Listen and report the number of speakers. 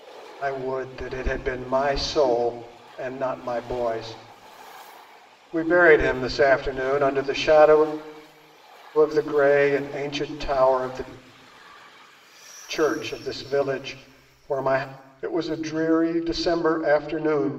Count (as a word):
one